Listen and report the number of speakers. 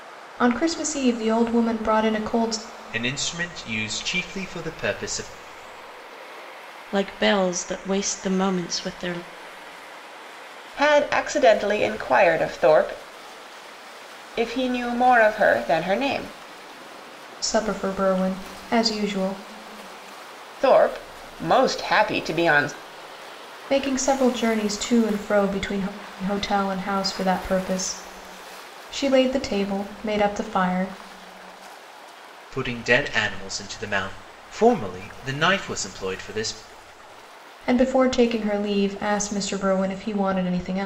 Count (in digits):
4